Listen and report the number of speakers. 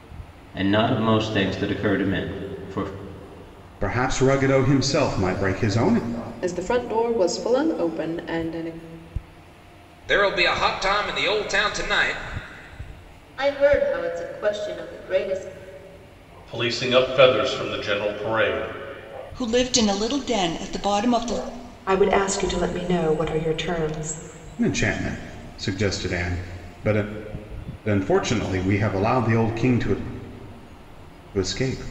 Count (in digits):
8